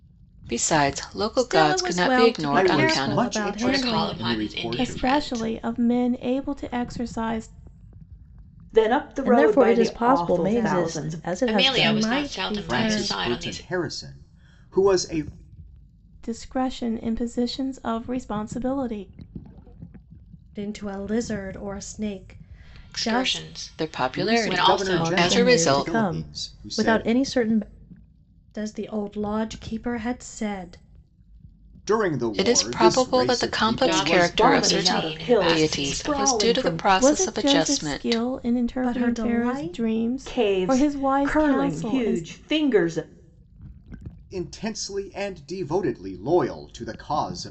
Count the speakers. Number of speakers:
seven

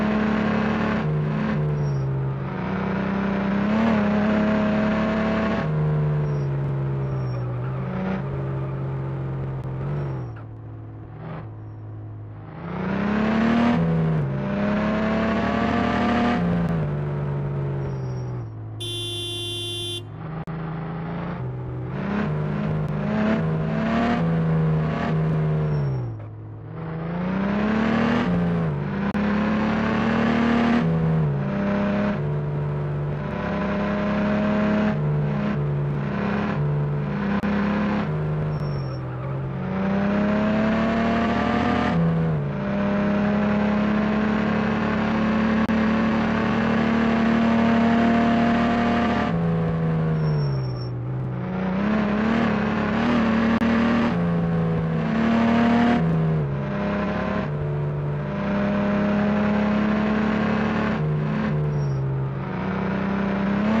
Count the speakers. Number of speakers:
zero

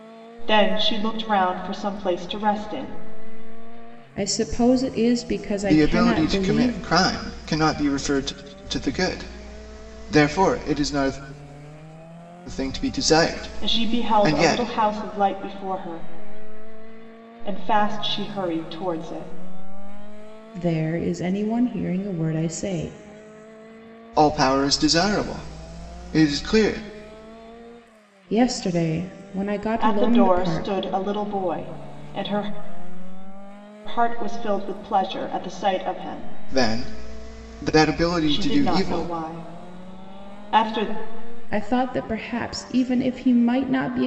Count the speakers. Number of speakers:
three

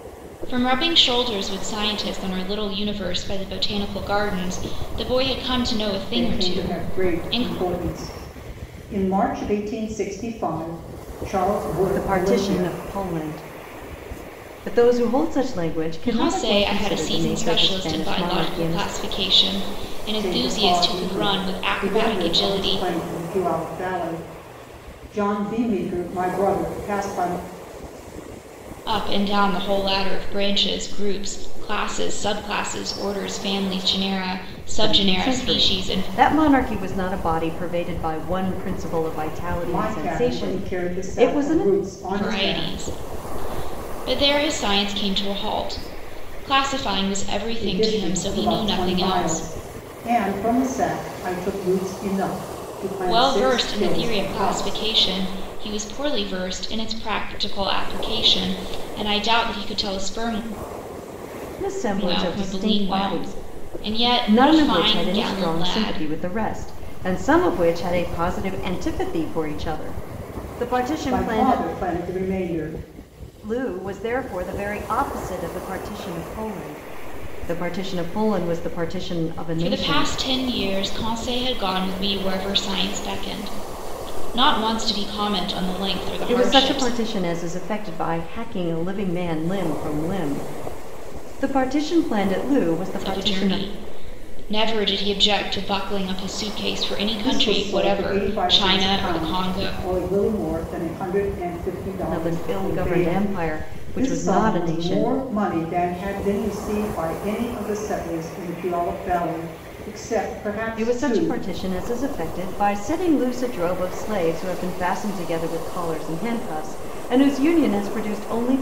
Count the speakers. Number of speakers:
three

